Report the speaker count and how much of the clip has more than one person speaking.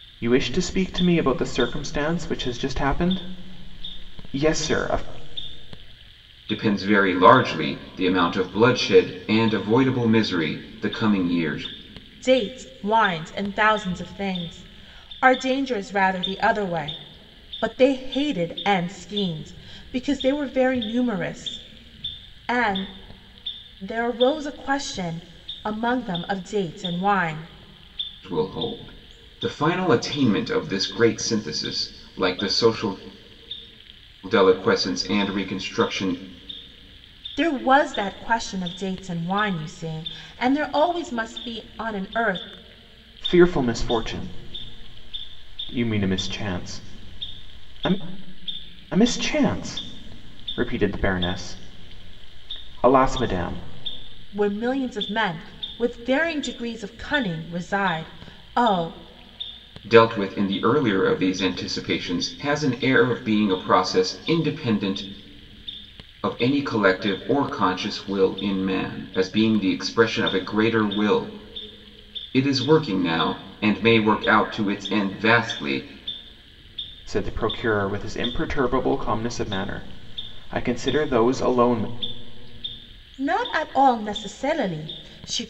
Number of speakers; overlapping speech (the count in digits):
3, no overlap